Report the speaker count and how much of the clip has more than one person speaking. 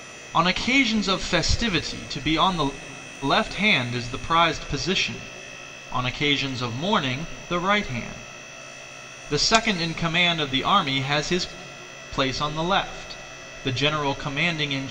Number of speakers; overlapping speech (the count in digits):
1, no overlap